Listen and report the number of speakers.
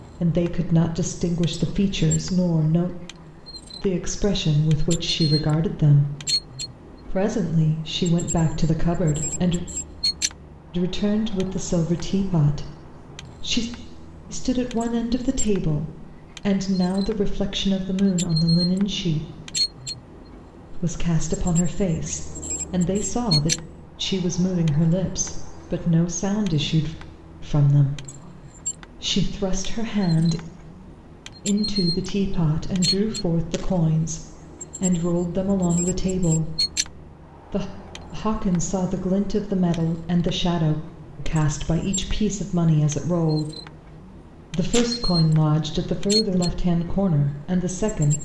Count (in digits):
1